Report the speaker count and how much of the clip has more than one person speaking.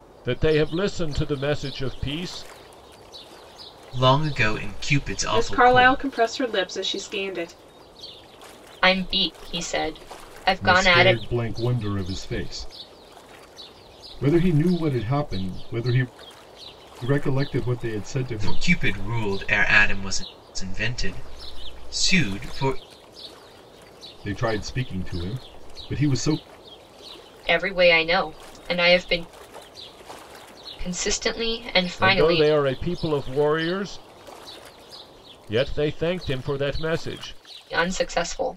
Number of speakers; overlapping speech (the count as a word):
five, about 6%